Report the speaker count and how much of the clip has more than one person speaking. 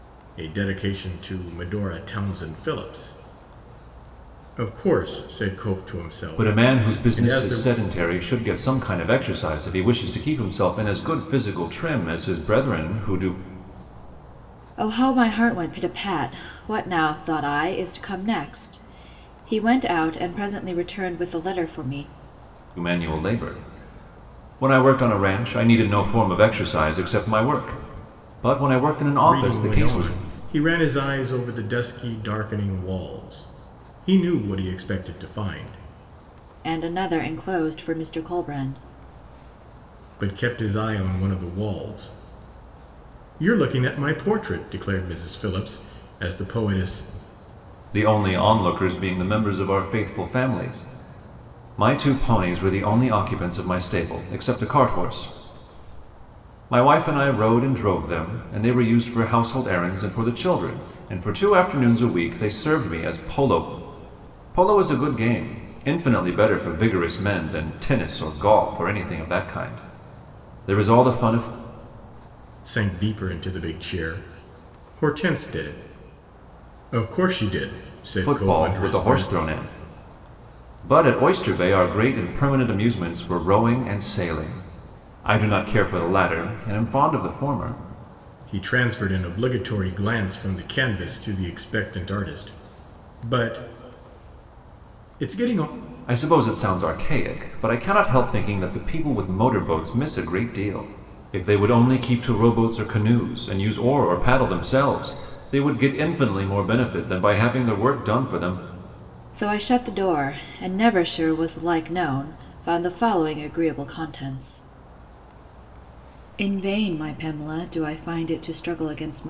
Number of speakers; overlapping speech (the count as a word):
three, about 3%